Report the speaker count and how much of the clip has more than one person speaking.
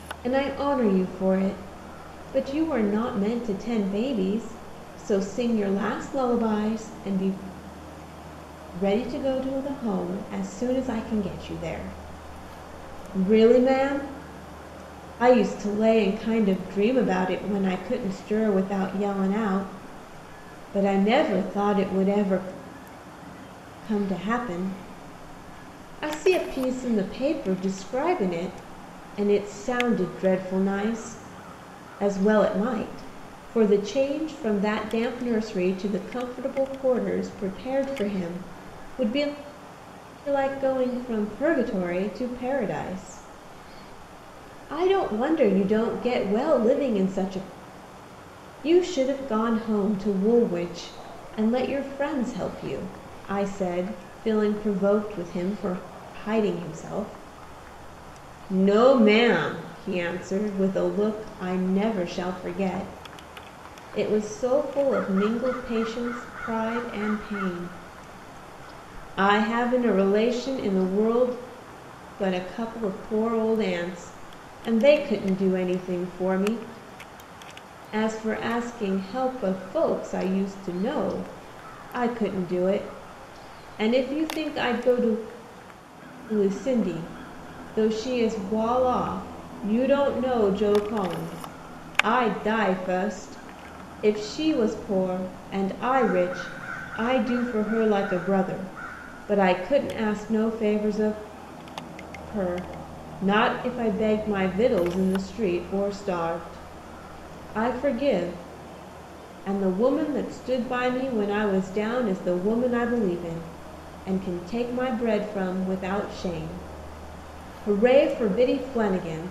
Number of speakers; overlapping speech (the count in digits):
1, no overlap